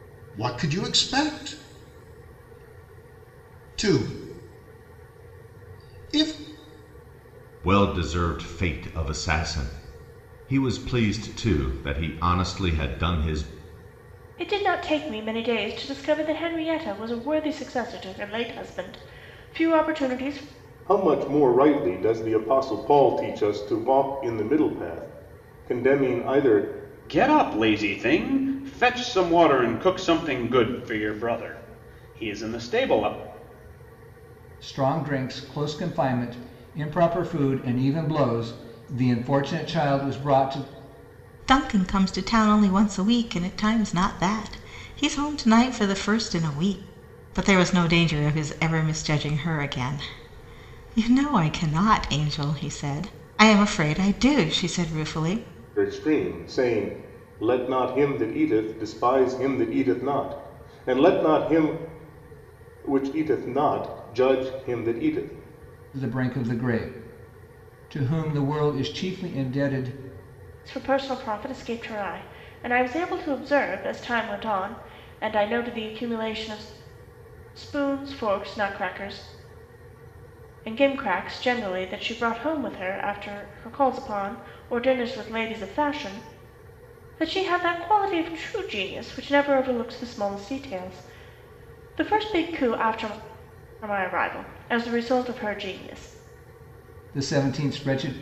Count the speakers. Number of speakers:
seven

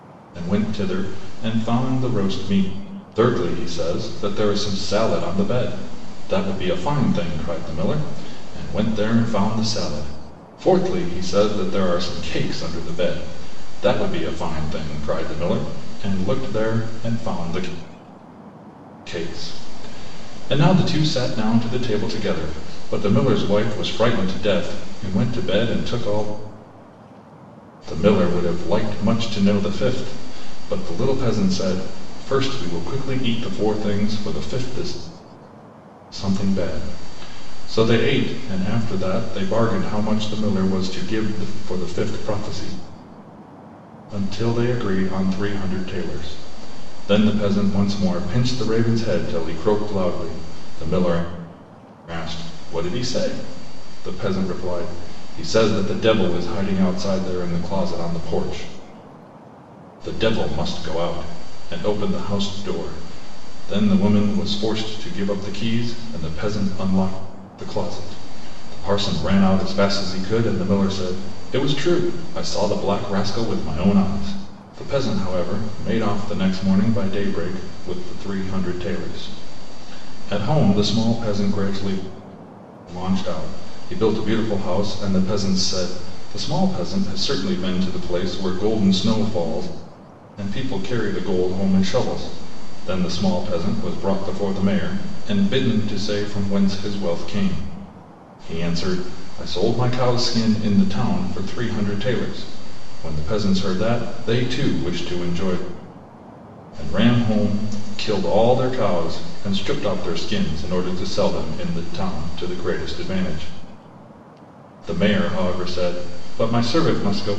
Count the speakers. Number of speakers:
one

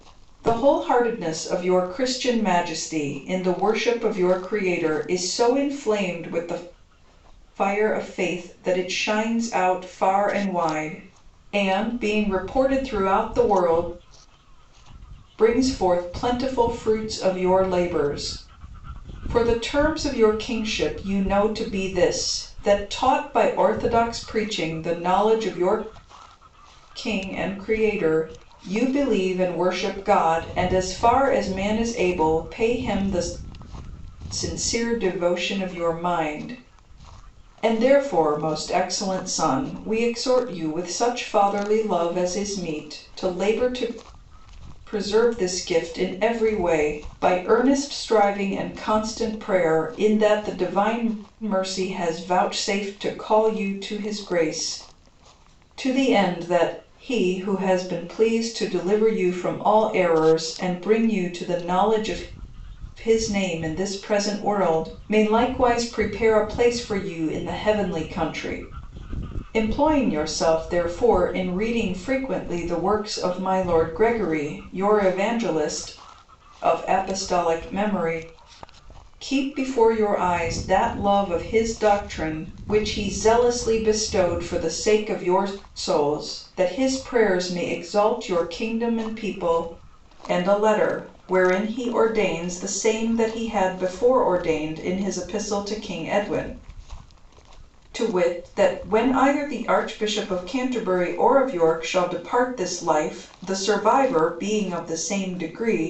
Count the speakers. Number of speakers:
one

